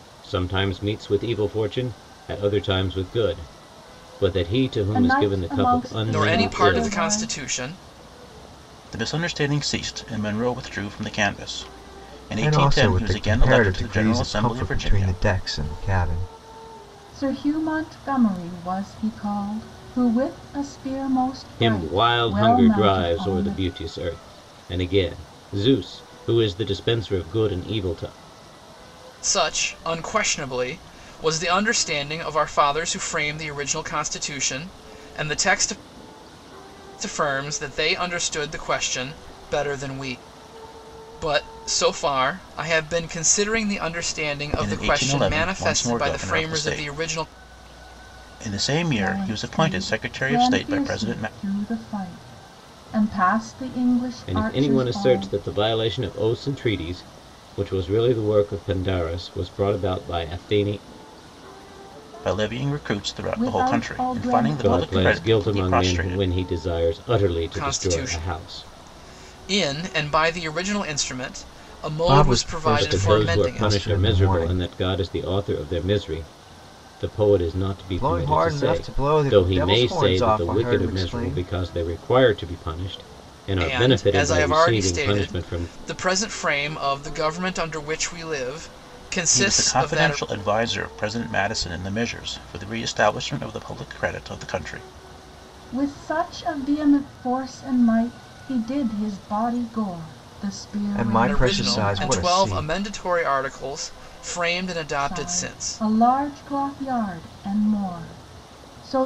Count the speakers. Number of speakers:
5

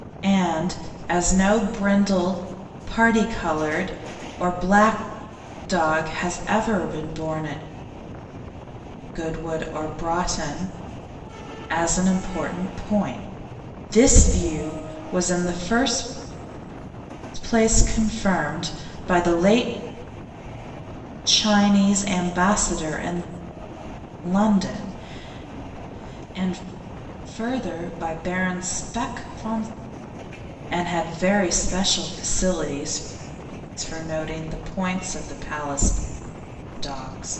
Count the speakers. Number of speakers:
1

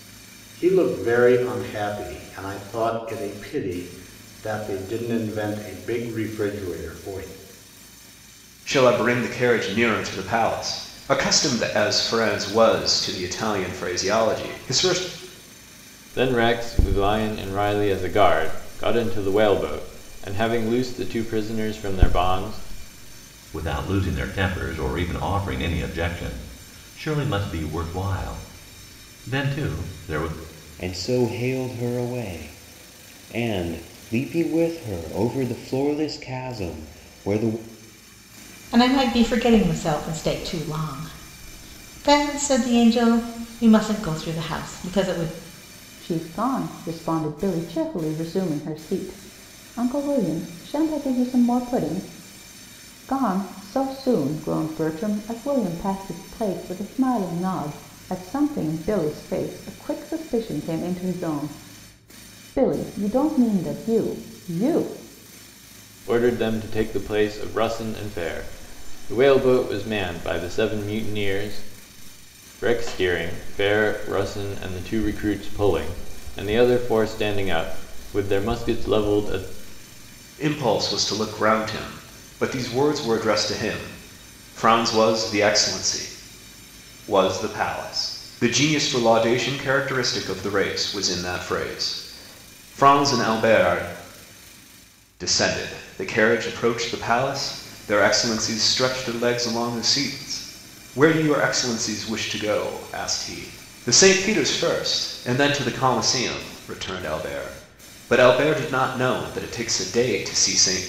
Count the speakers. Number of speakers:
7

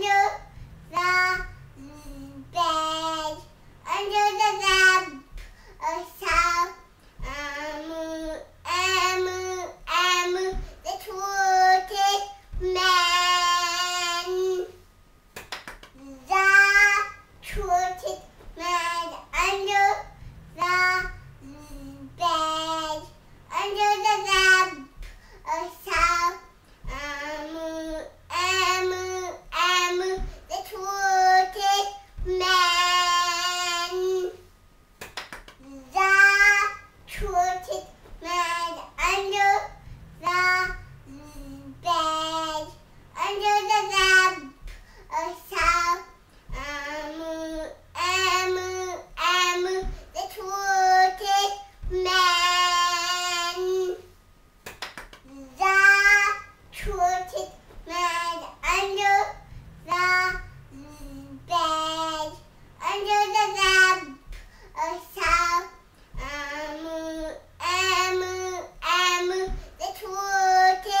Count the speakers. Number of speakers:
0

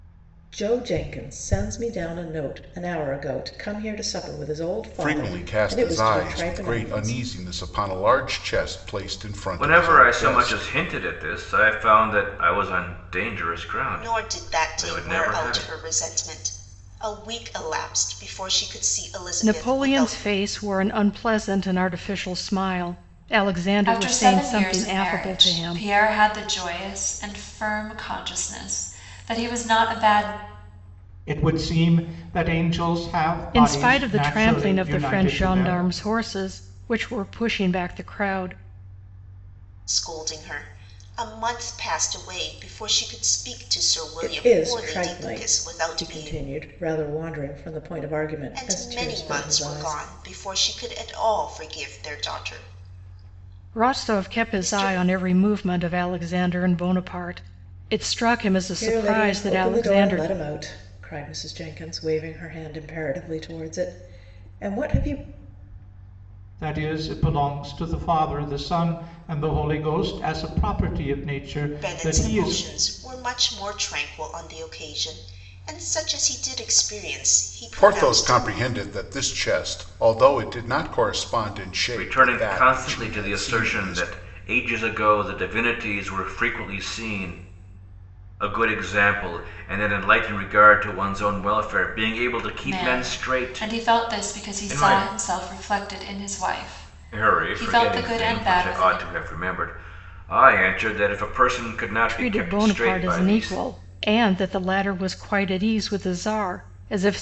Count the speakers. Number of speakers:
7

